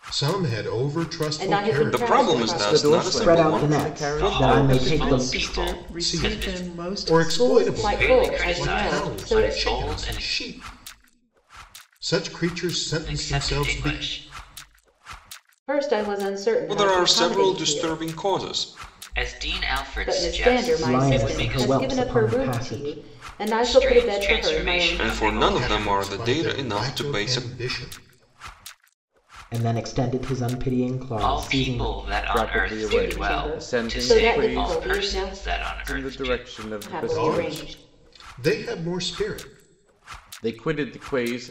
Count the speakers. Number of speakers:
seven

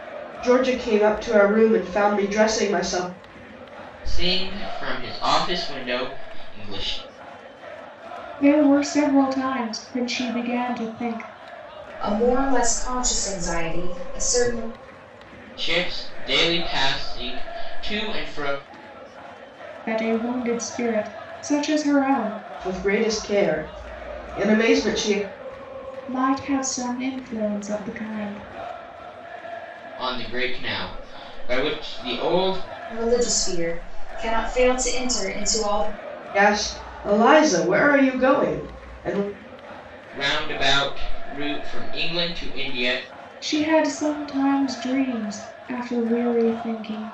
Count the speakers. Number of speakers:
four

